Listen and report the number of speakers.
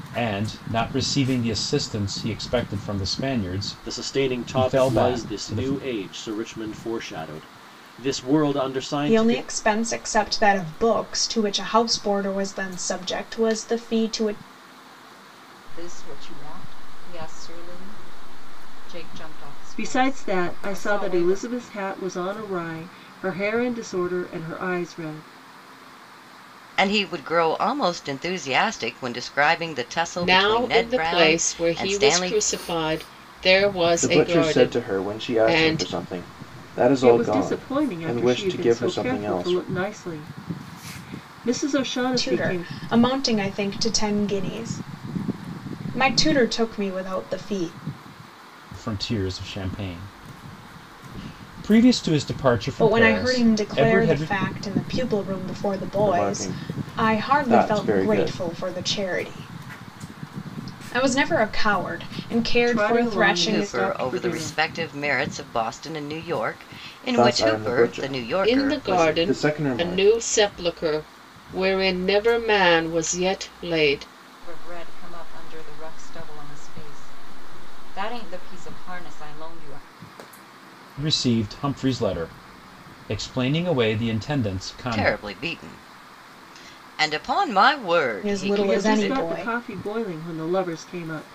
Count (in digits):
8